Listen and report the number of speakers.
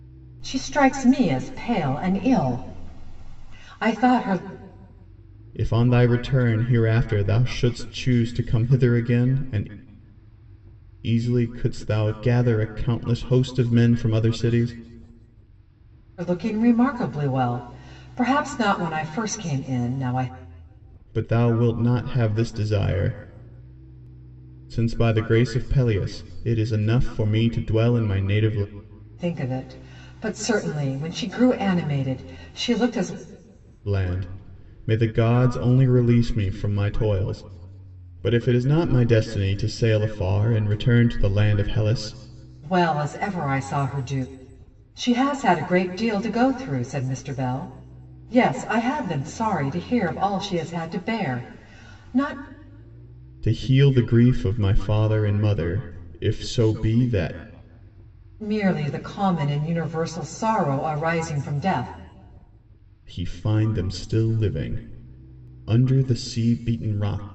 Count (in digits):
2